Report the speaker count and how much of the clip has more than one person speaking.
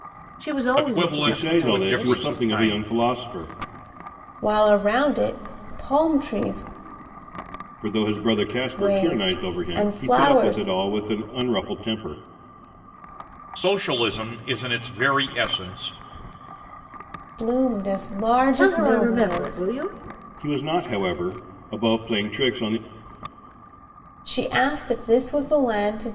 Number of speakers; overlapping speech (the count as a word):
four, about 20%